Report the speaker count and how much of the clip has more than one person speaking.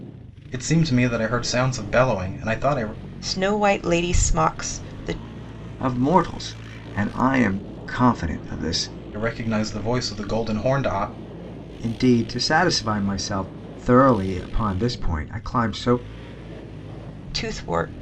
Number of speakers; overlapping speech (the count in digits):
3, no overlap